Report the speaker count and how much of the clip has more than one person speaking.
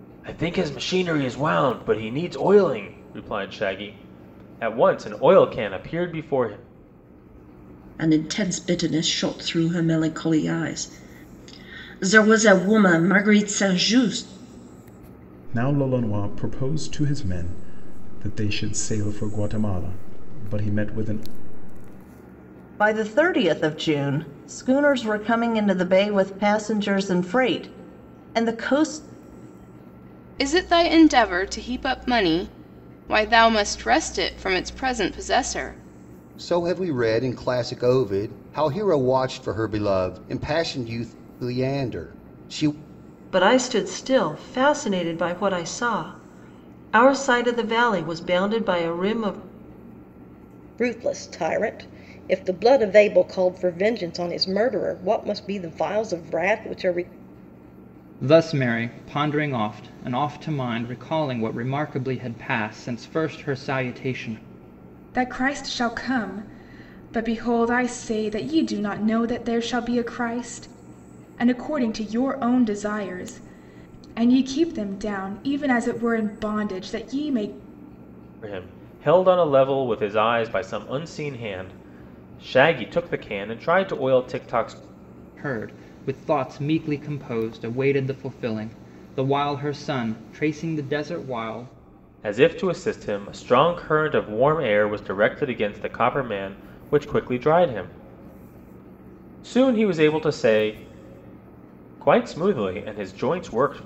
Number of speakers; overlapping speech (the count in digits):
10, no overlap